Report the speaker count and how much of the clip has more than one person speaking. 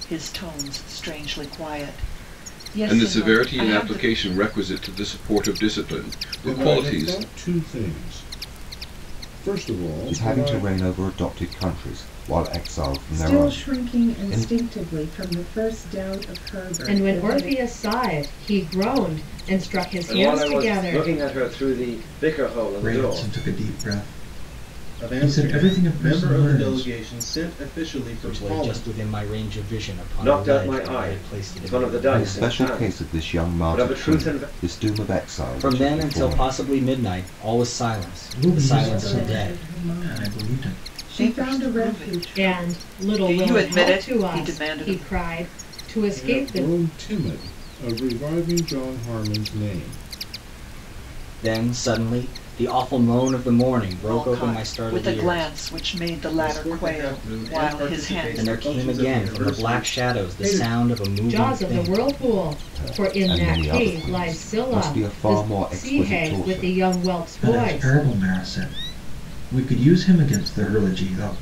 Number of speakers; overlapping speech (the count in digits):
10, about 46%